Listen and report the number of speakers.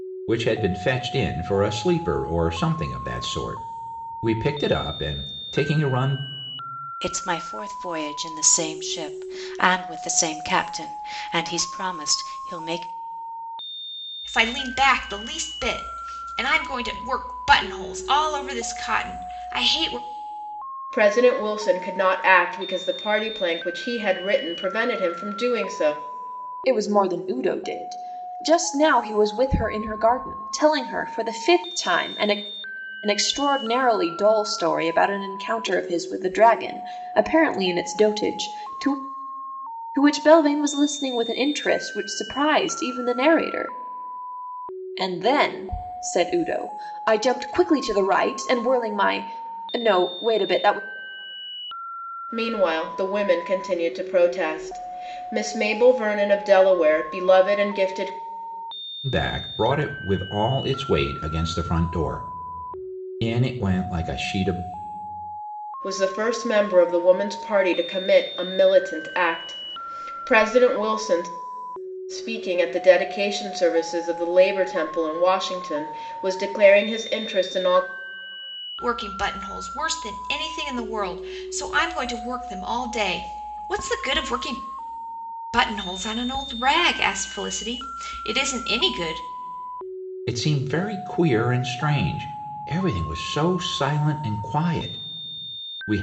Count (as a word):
five